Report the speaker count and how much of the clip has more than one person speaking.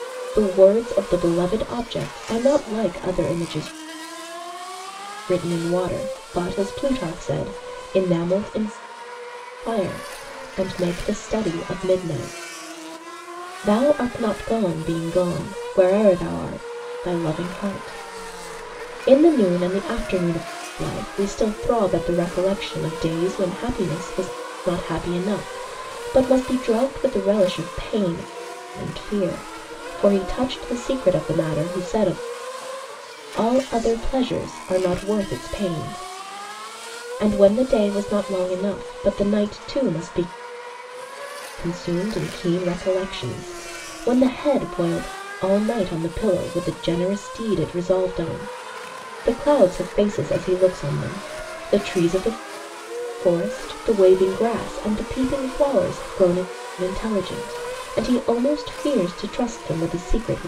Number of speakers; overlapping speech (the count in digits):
1, no overlap